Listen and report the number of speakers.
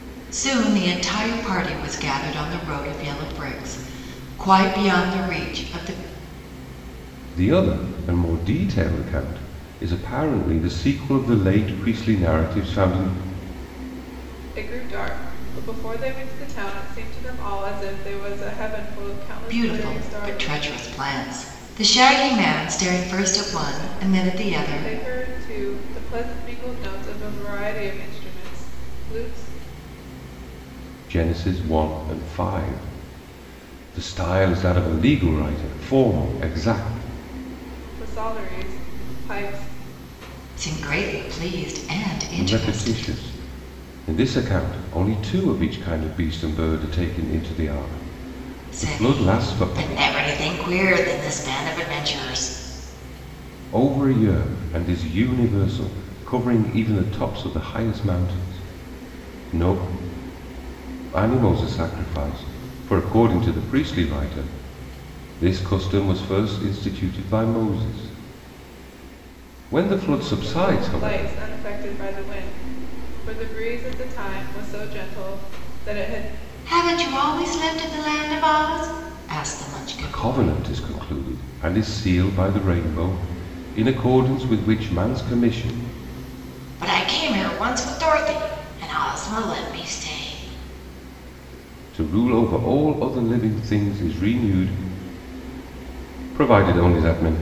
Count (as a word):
three